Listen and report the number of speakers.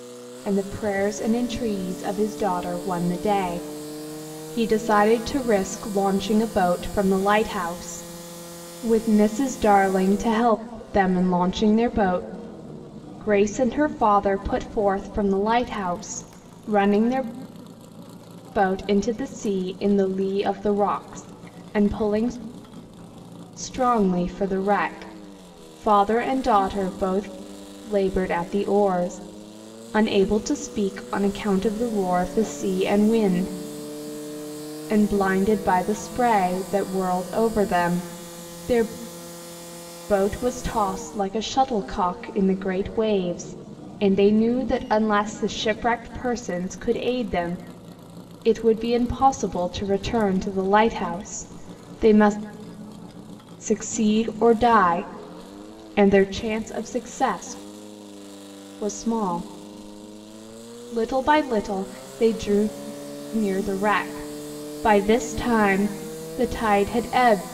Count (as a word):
one